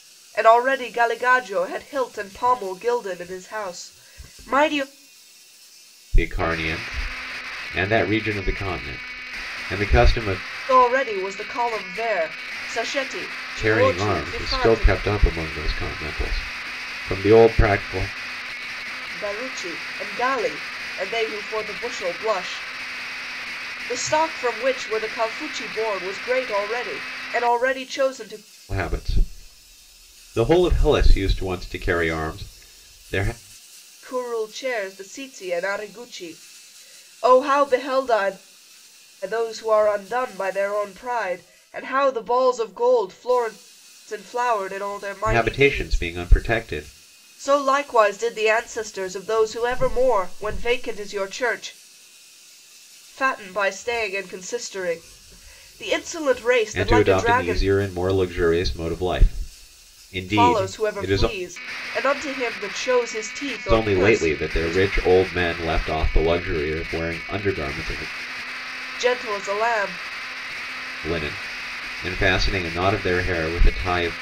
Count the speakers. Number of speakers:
2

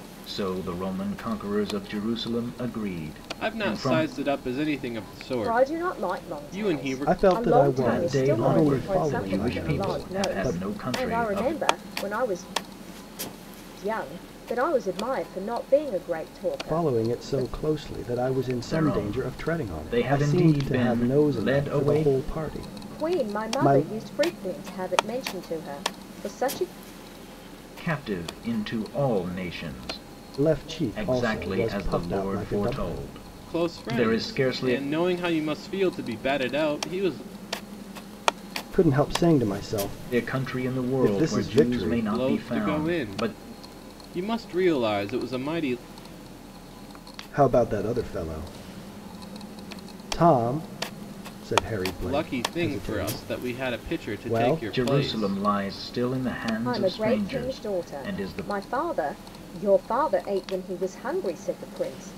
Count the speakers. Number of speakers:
4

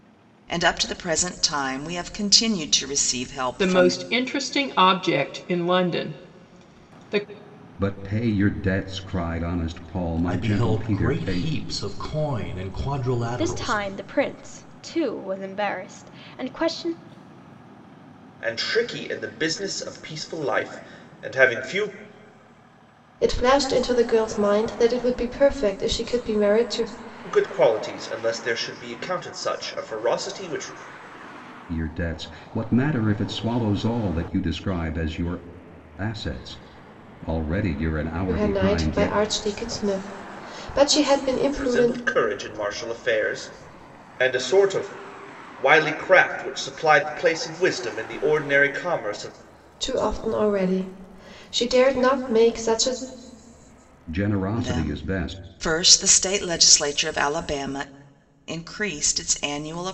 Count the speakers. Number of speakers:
7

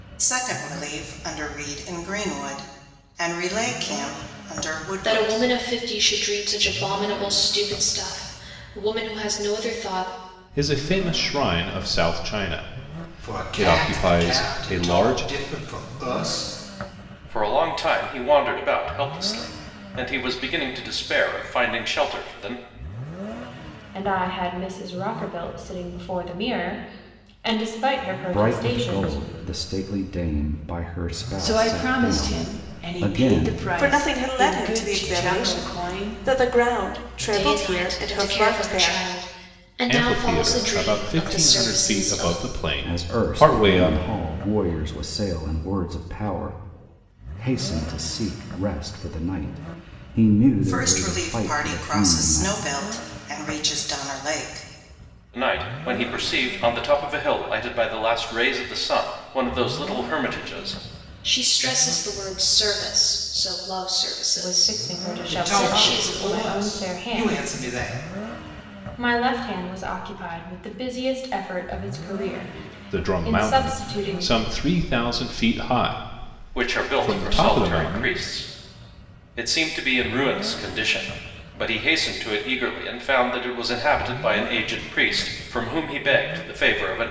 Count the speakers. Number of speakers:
9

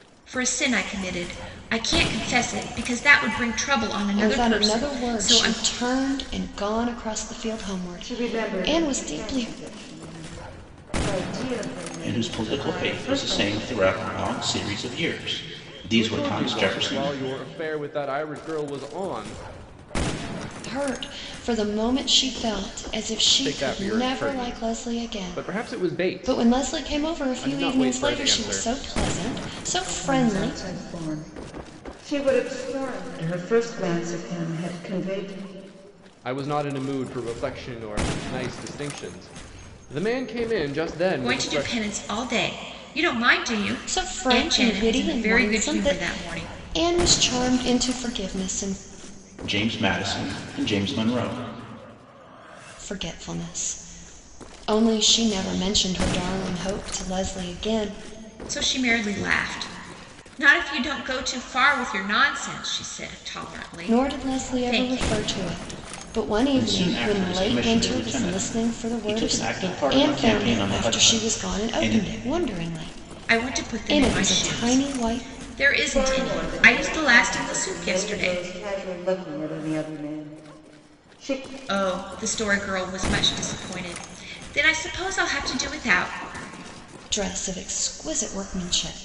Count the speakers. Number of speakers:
5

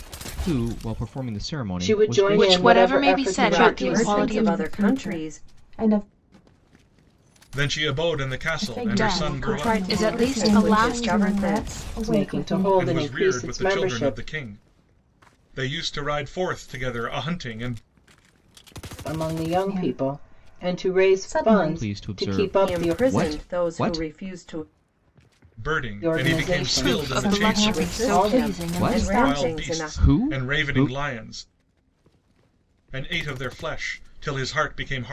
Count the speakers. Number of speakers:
6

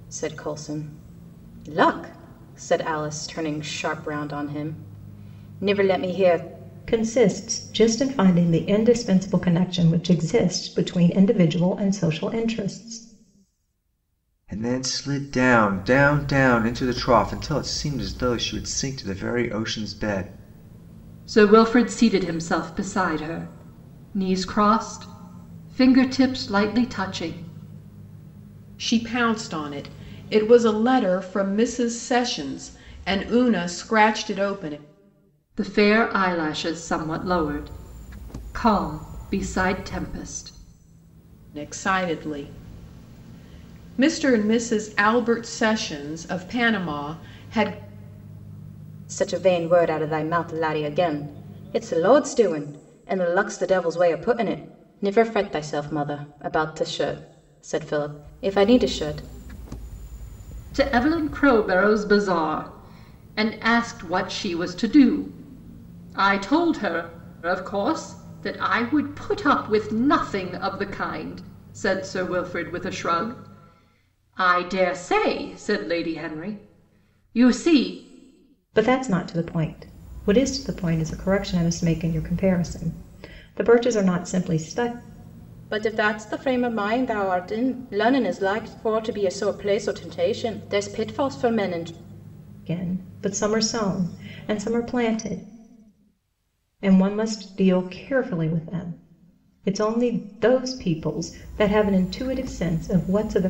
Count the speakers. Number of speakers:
5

